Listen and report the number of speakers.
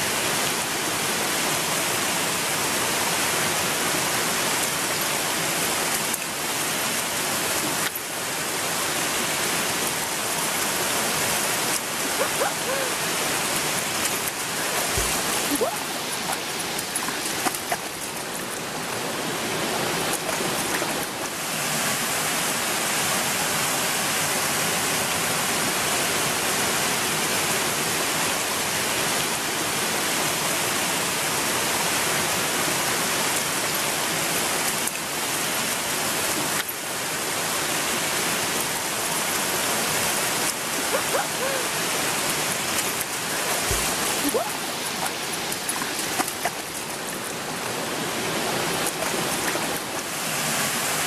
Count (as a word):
zero